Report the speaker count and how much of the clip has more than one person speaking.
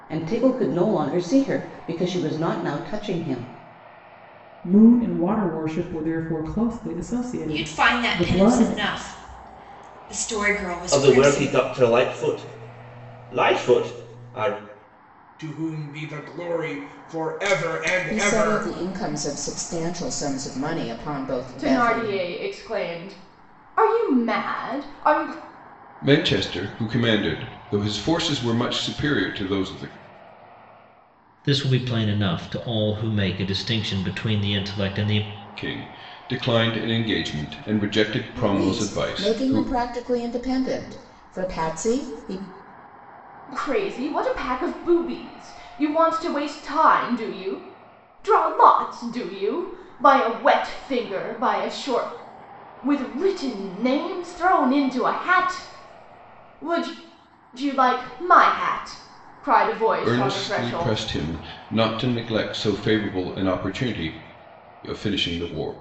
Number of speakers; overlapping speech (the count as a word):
nine, about 8%